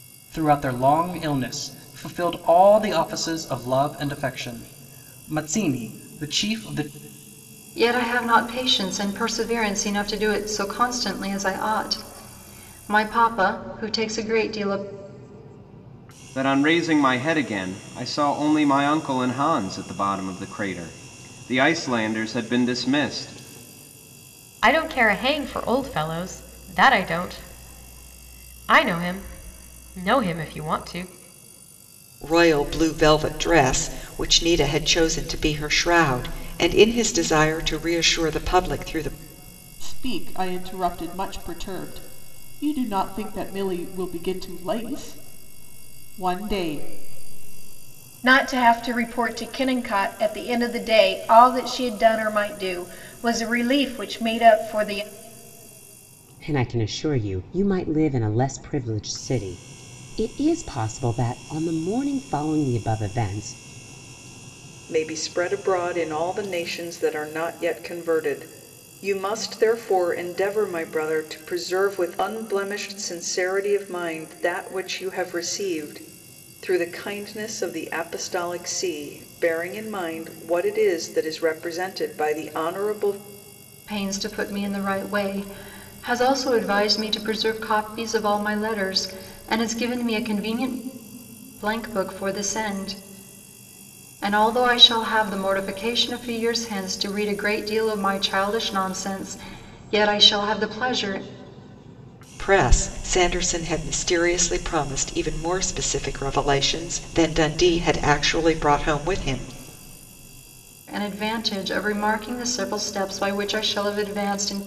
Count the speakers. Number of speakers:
nine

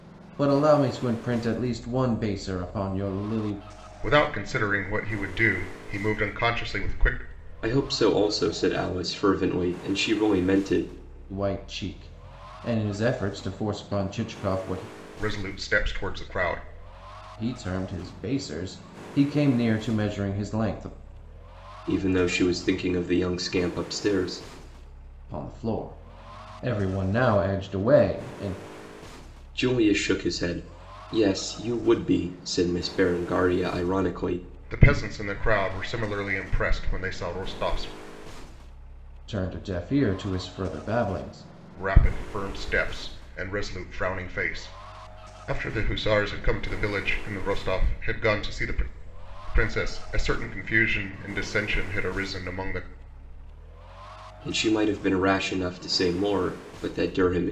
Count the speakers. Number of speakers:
three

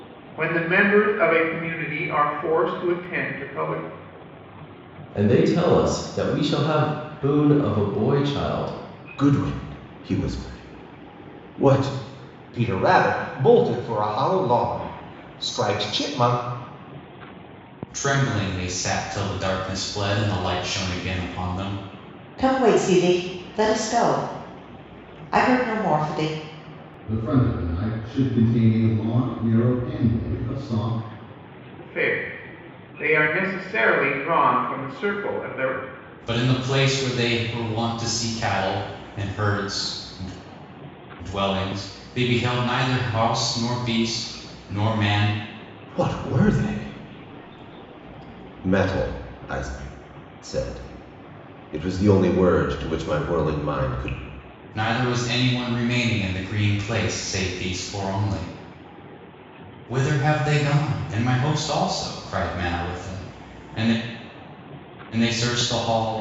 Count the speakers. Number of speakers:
seven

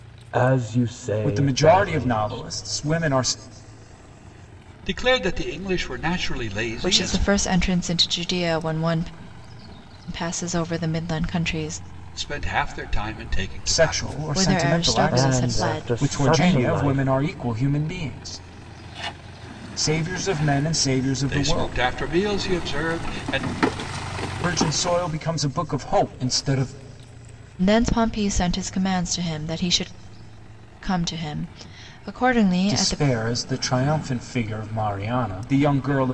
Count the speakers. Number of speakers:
four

